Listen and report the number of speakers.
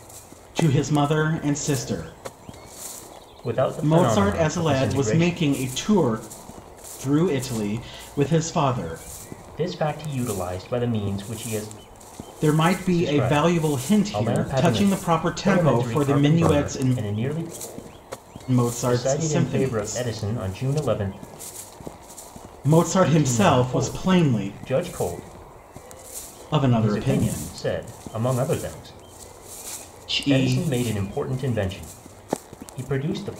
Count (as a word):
two